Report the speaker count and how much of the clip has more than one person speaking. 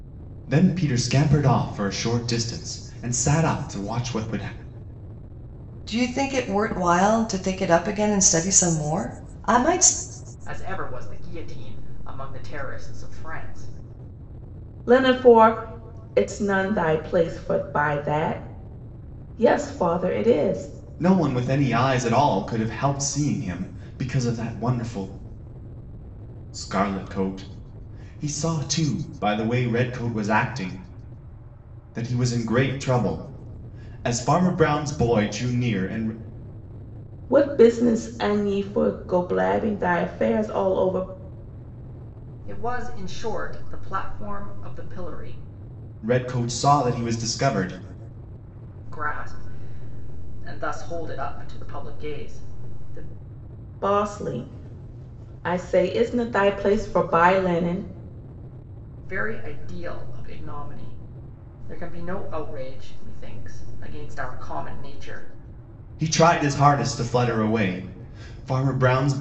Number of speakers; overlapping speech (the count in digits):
4, no overlap